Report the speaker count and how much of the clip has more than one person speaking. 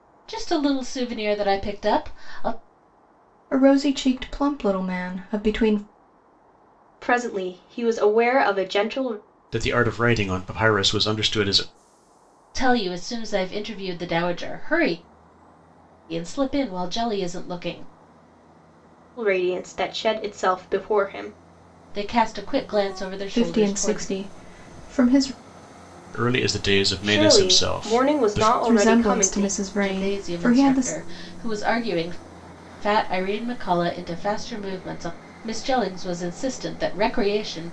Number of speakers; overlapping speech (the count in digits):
4, about 12%